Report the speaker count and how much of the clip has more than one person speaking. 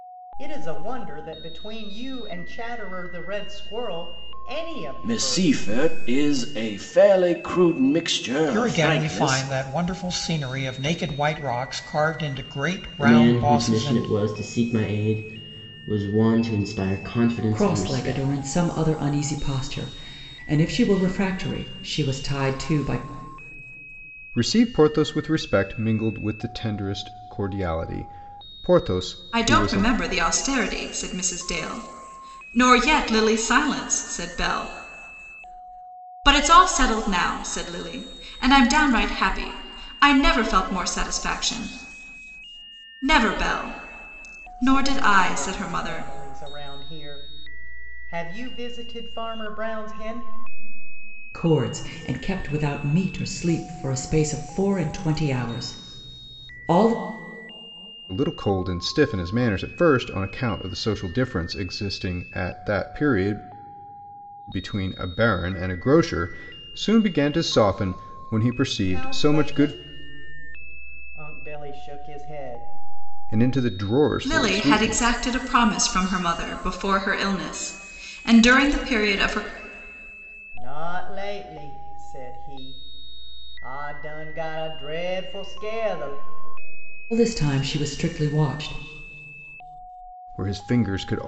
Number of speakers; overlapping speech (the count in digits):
7, about 9%